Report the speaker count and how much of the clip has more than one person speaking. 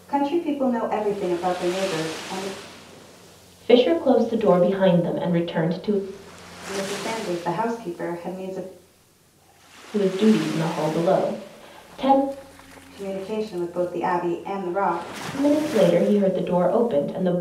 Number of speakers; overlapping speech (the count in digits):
2, no overlap